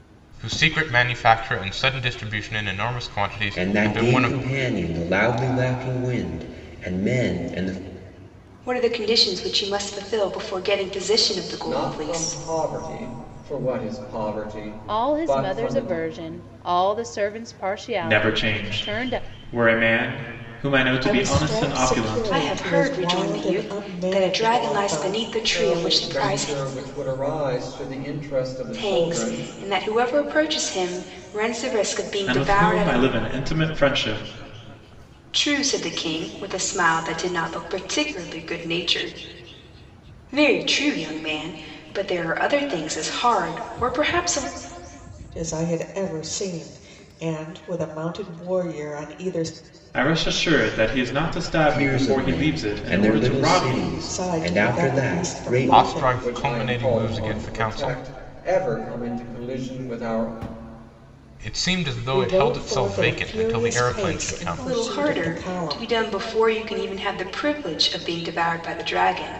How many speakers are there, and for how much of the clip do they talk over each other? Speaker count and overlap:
7, about 30%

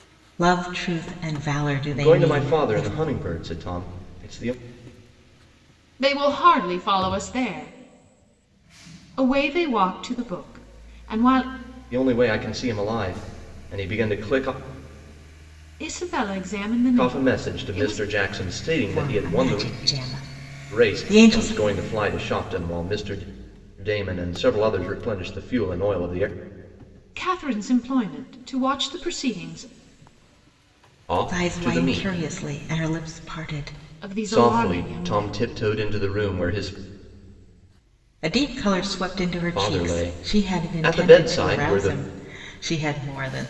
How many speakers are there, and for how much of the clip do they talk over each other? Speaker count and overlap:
3, about 20%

